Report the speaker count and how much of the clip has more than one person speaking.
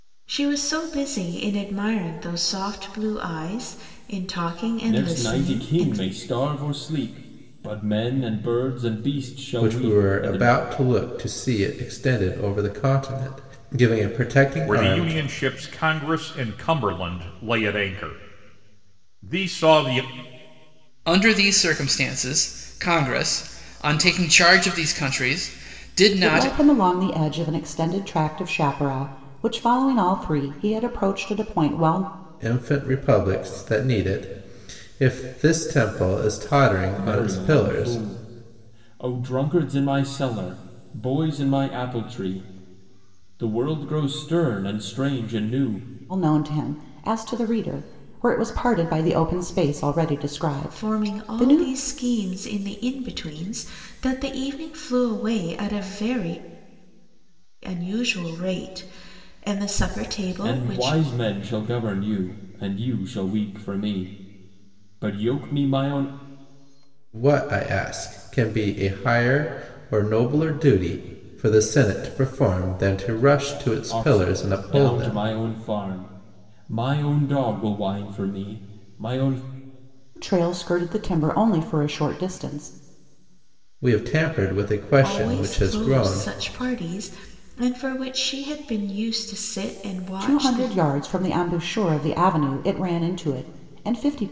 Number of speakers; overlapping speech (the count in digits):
6, about 10%